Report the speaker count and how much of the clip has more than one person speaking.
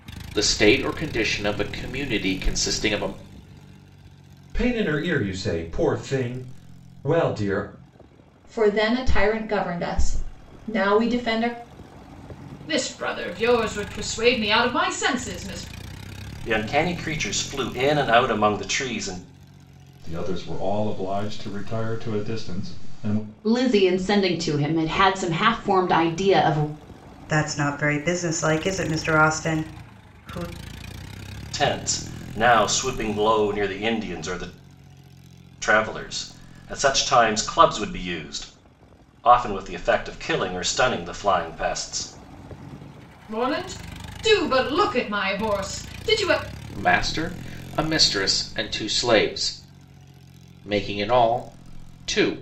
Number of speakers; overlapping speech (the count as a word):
eight, no overlap